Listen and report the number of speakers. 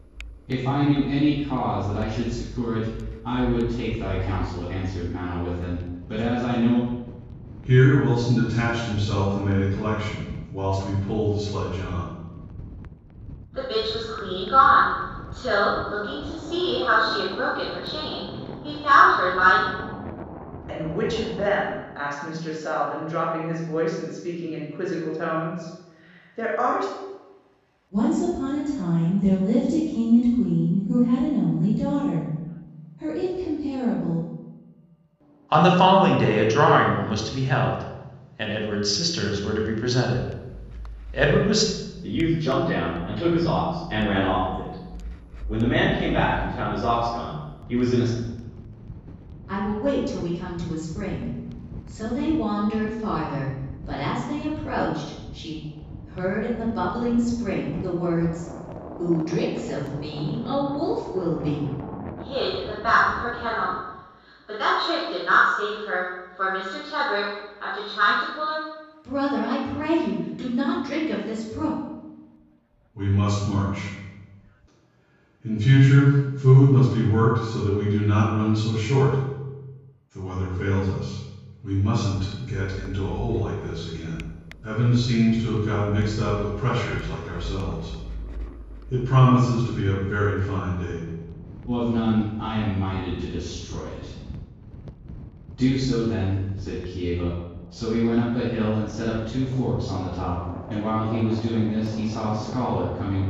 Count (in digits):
8